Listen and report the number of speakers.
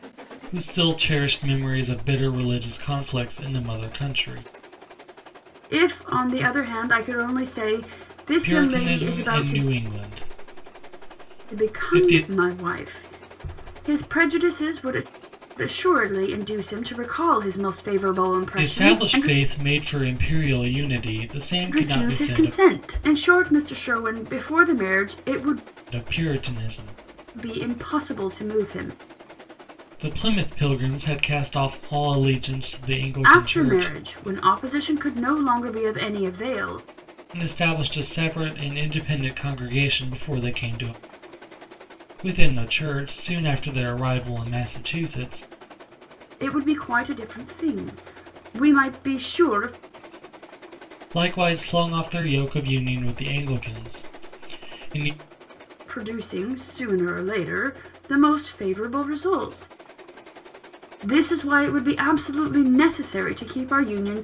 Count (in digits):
2